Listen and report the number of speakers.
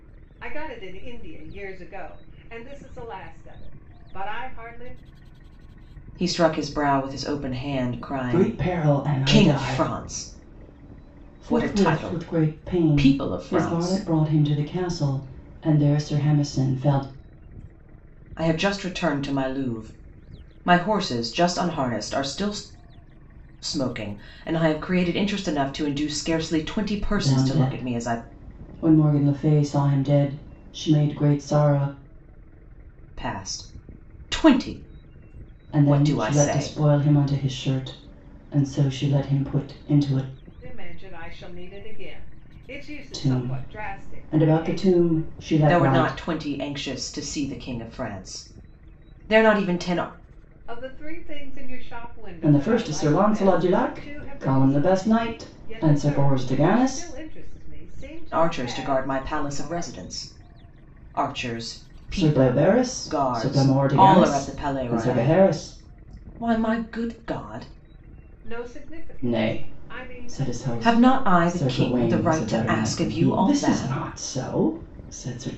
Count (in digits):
3